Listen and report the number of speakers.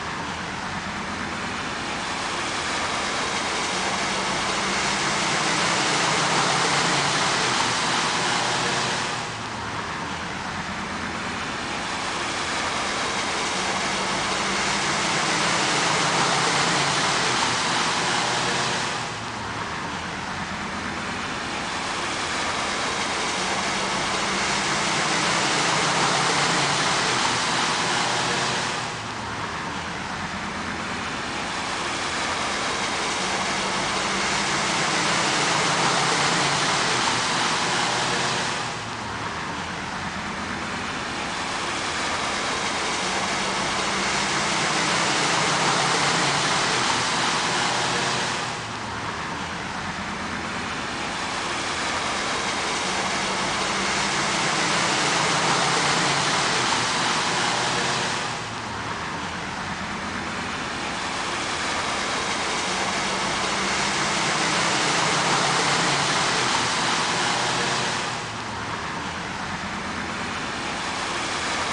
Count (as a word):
zero